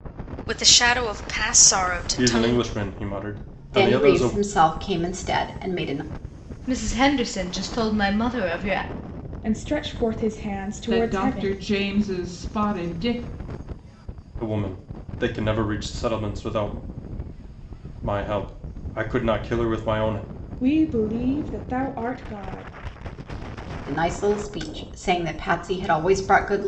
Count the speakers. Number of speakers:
6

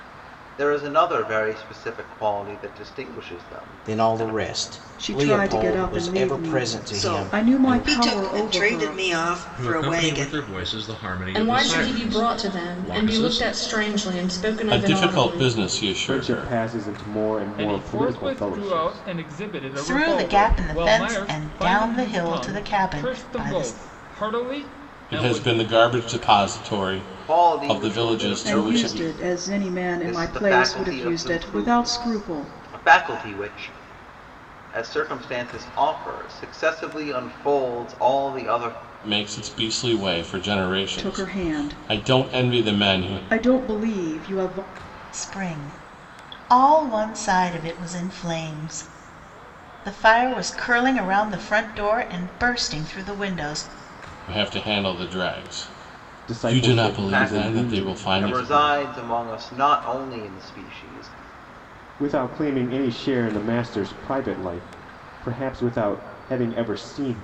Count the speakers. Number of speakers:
10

